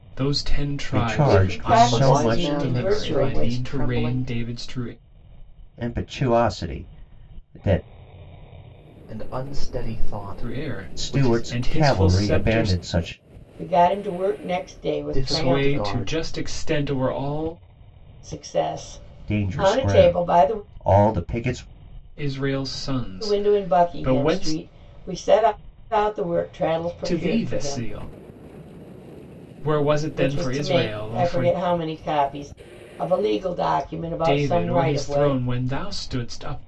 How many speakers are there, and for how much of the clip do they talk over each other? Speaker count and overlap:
four, about 36%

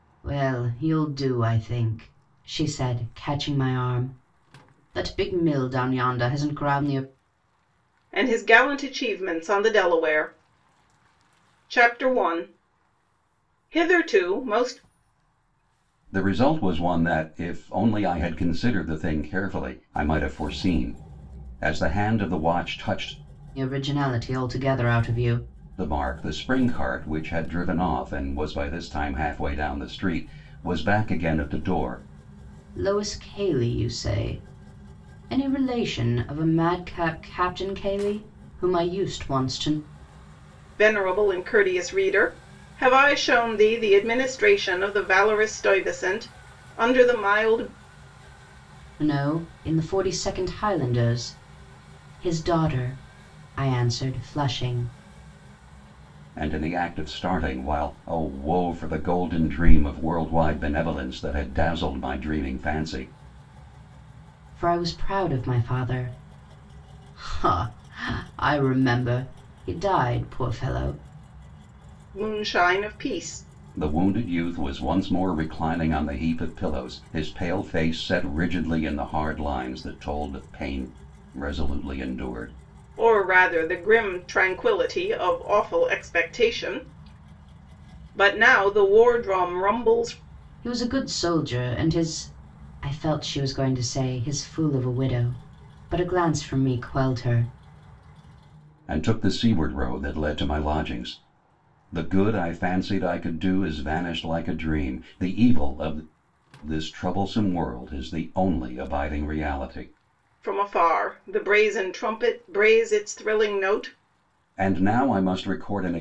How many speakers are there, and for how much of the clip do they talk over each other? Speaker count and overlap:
three, no overlap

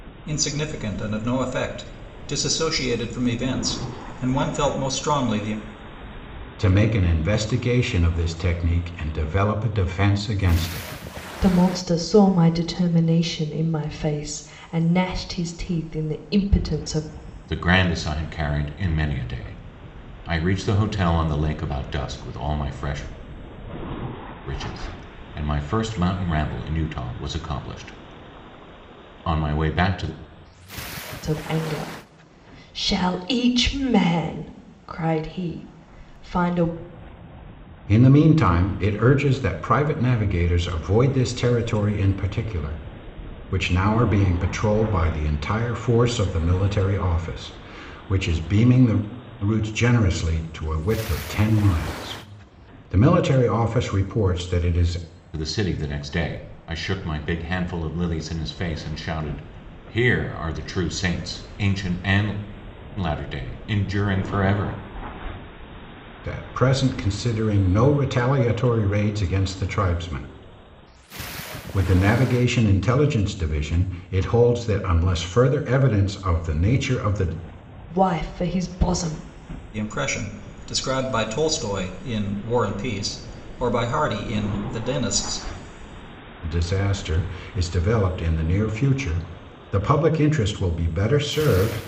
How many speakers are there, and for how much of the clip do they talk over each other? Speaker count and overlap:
four, no overlap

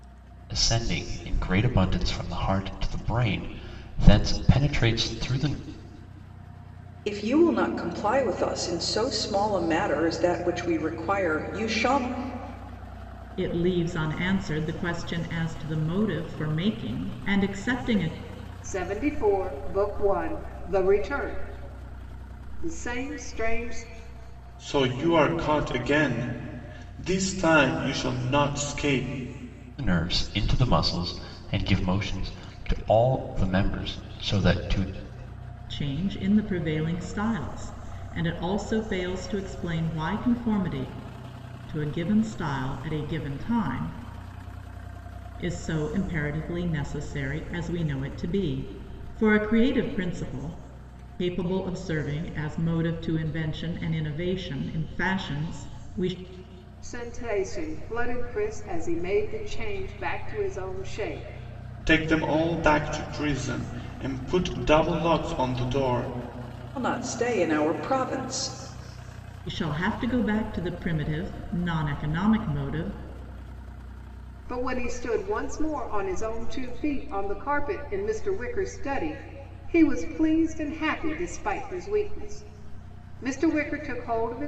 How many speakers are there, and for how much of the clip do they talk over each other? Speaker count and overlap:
five, no overlap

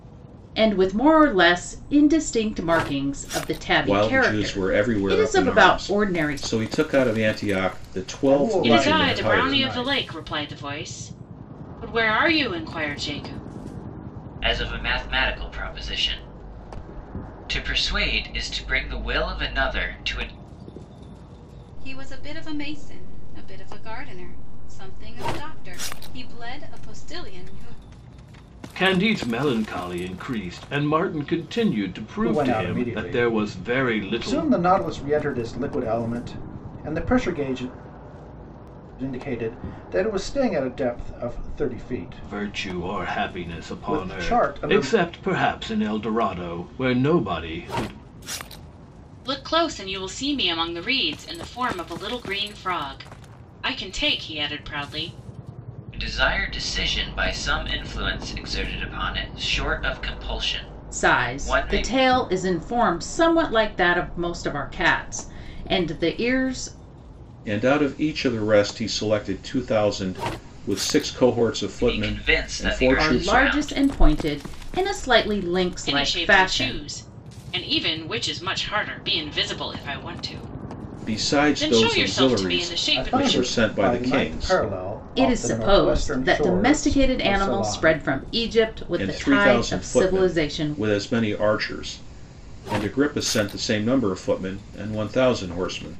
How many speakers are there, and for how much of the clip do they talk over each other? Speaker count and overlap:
seven, about 23%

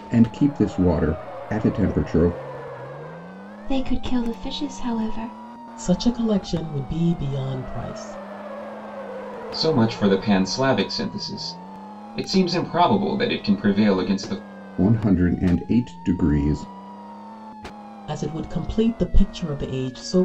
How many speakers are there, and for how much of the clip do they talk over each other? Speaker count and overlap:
four, no overlap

